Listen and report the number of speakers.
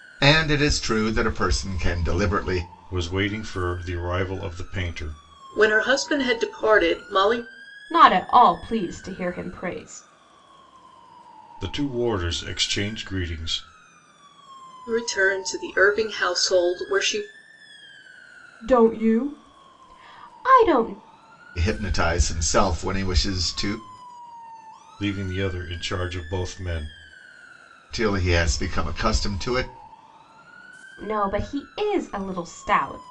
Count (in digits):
4